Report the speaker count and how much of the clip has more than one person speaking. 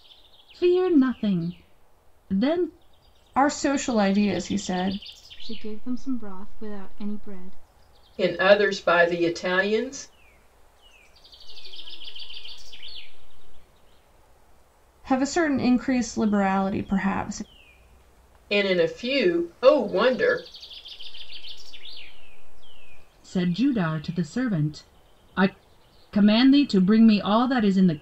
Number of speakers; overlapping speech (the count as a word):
five, no overlap